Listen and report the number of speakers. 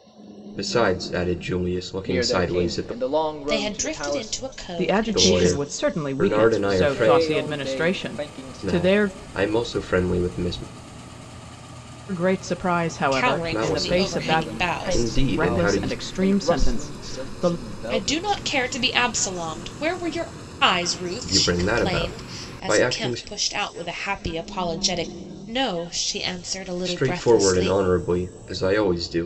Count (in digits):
4